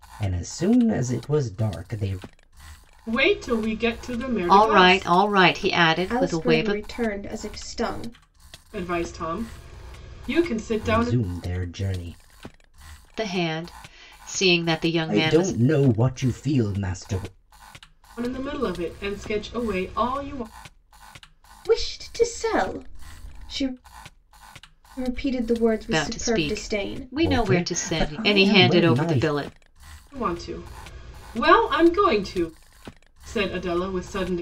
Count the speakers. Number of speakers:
4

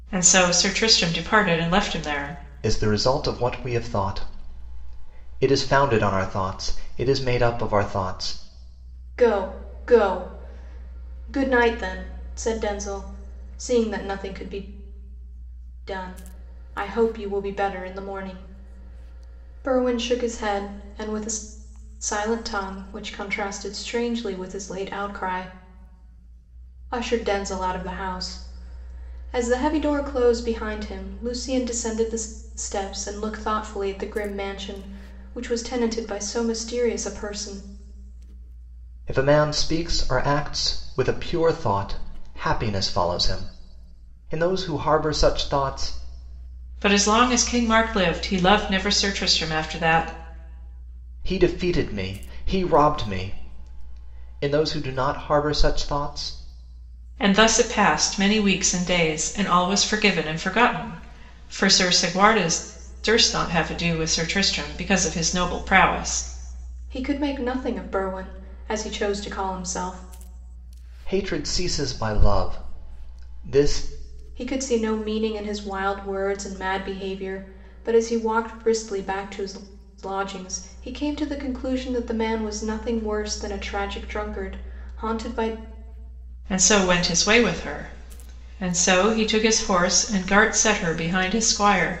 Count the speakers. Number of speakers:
3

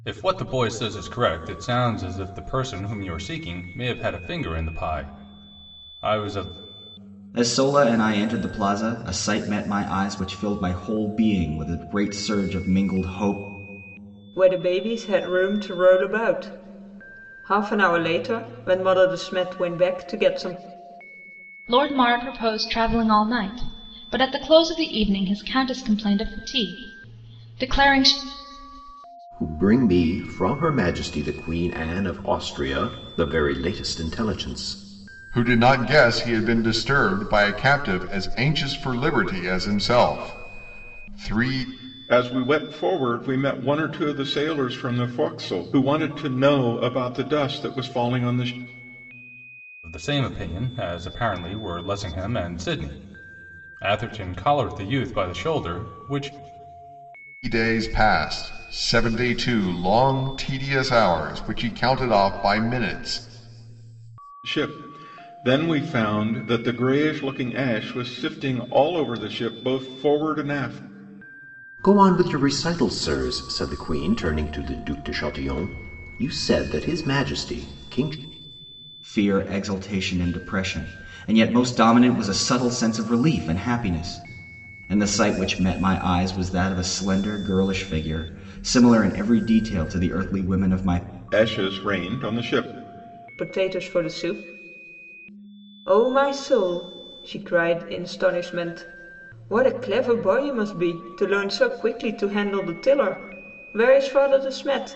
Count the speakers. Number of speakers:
7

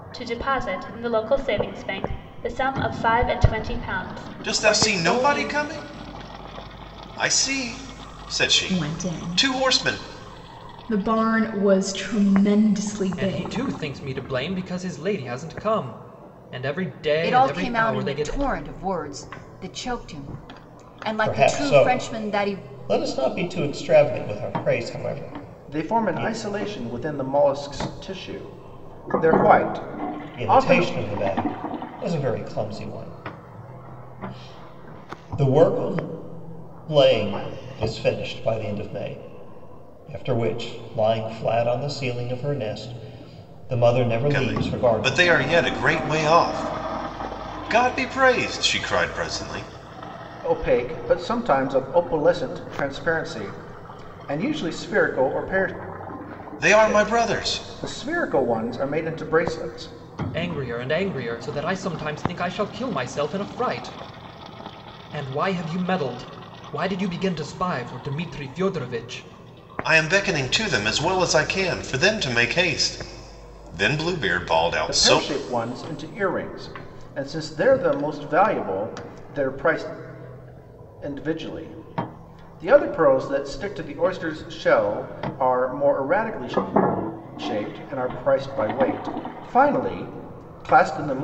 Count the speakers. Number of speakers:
7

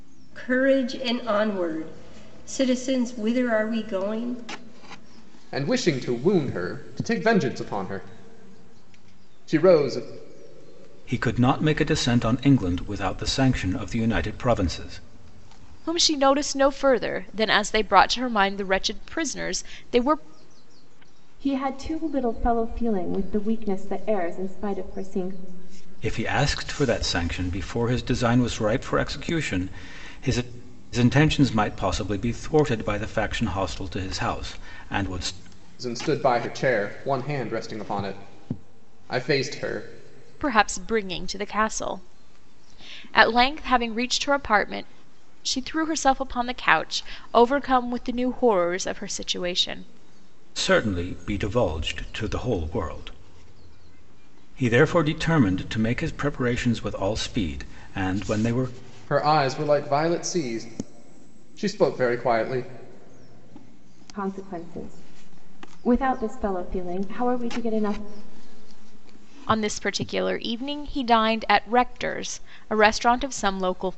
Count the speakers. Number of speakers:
5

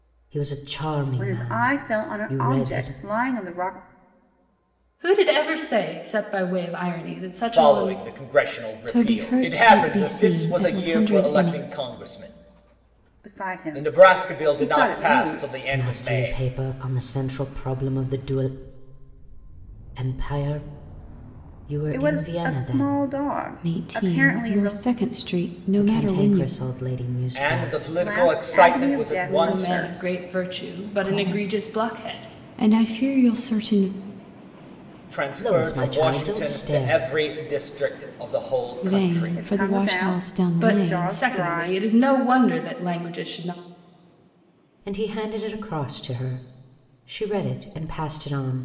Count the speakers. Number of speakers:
5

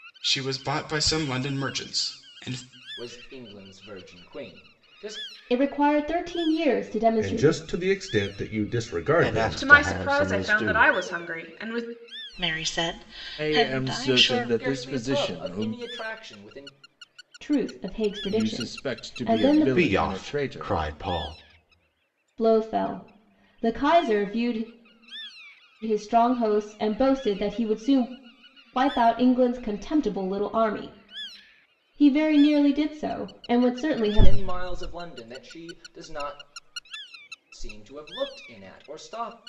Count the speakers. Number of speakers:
8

